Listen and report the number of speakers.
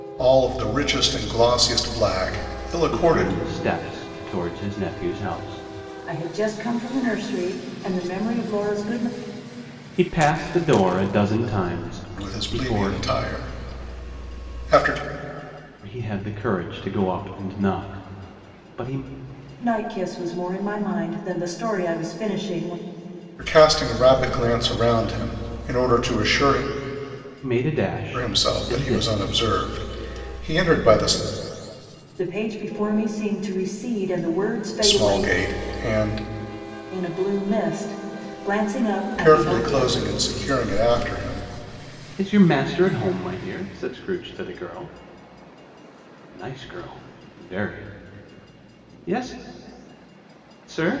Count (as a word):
three